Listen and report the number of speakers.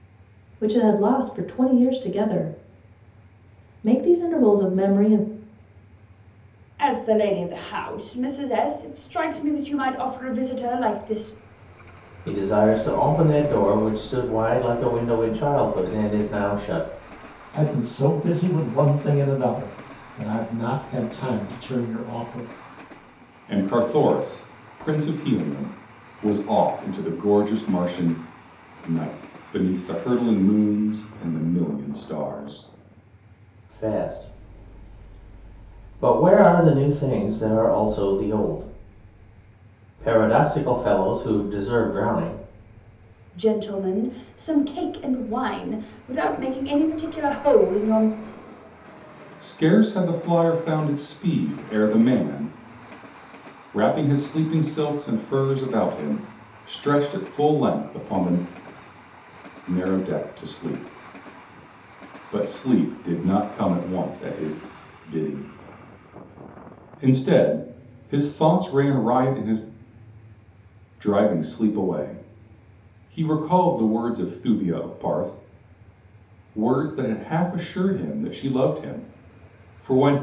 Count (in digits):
5